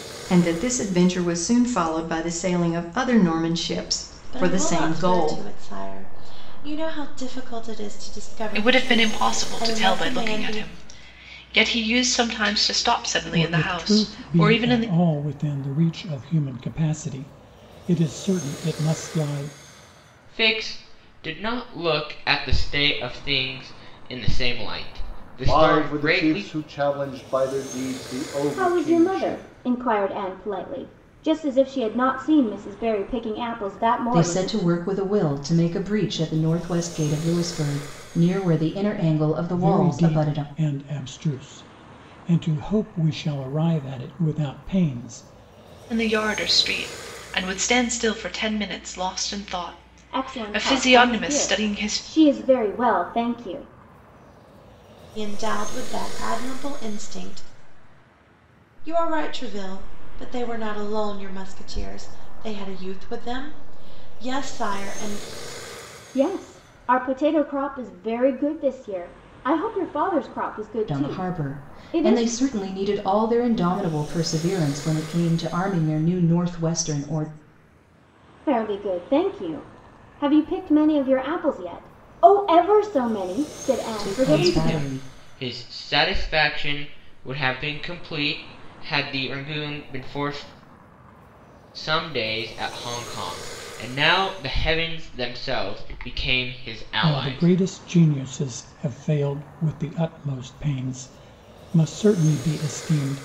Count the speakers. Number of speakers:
8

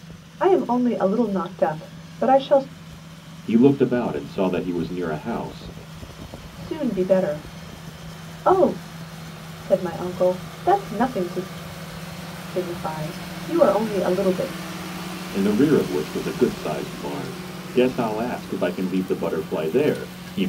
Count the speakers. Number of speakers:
2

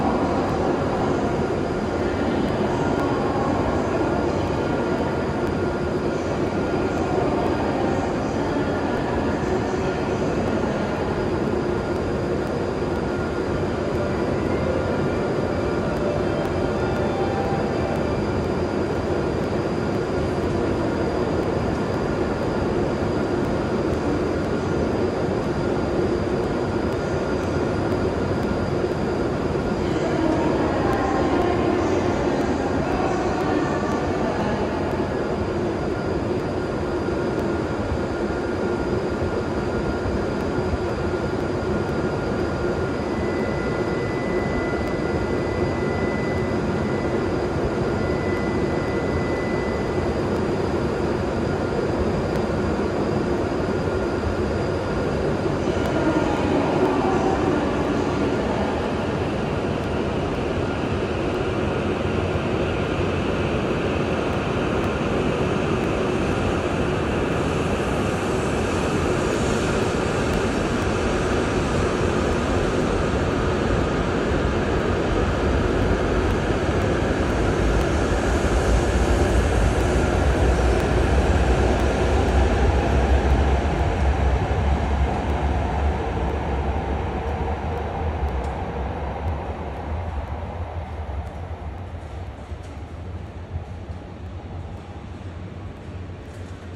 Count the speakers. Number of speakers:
0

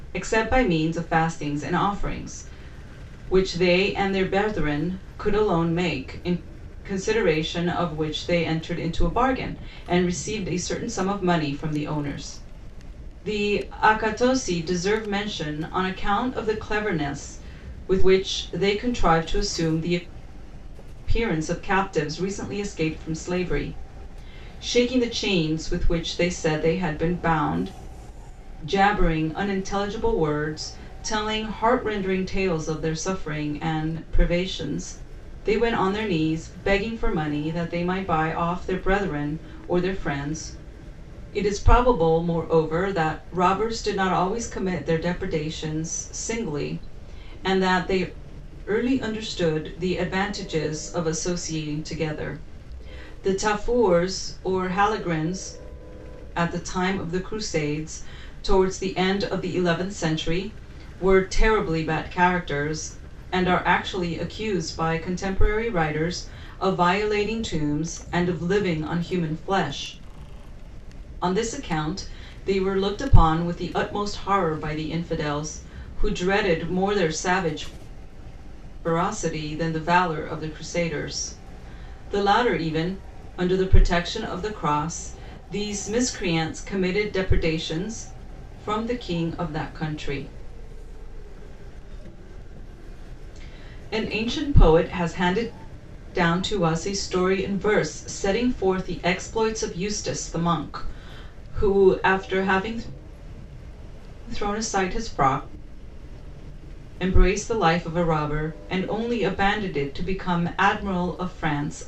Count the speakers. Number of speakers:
1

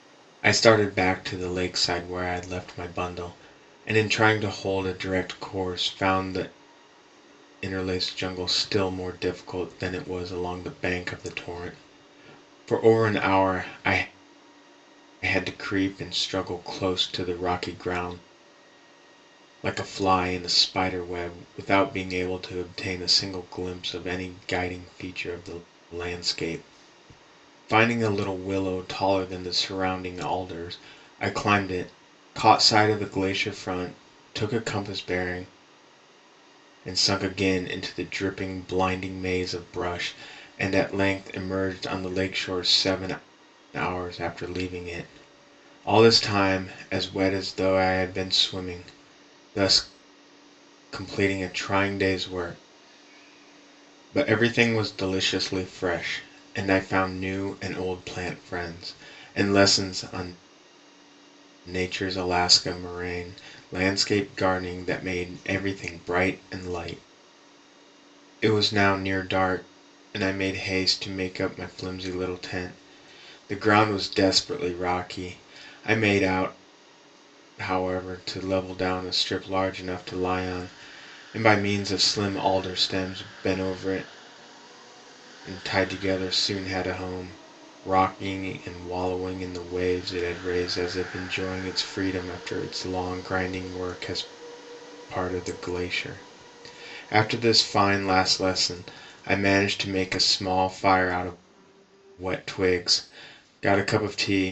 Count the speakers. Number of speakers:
1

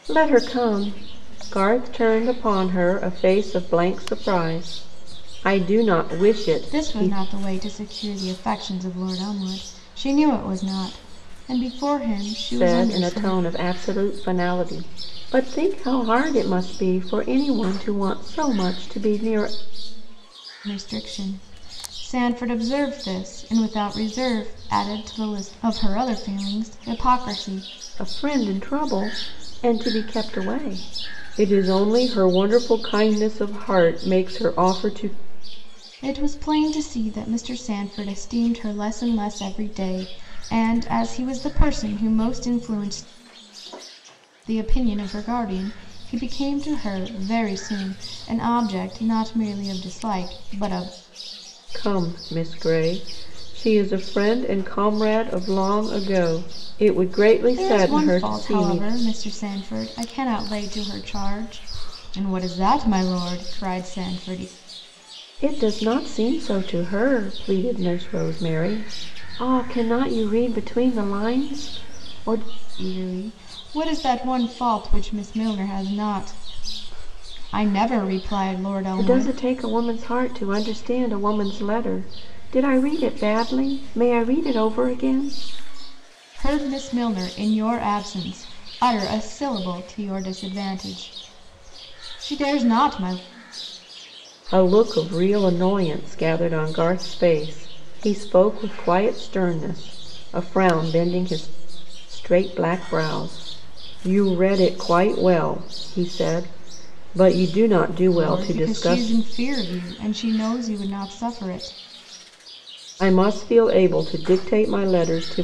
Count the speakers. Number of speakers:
2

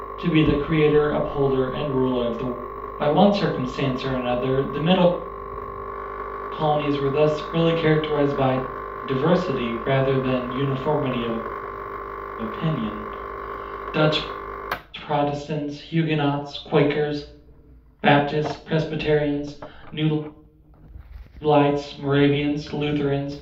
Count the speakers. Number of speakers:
1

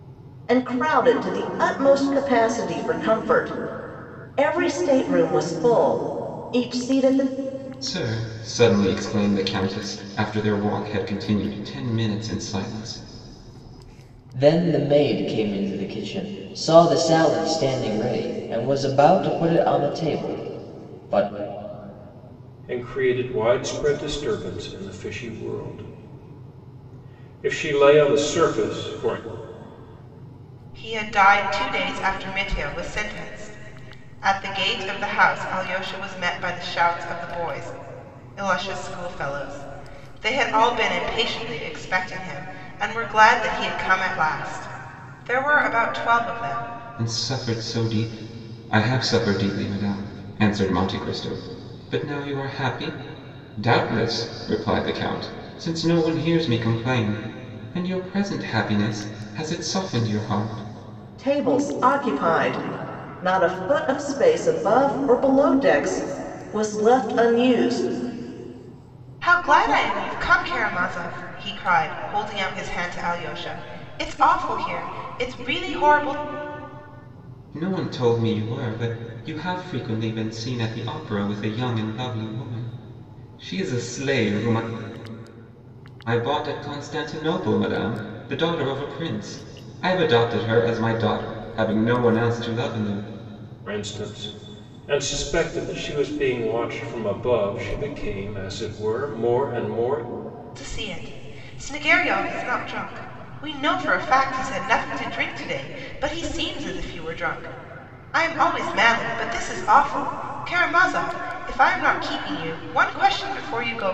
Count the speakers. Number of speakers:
5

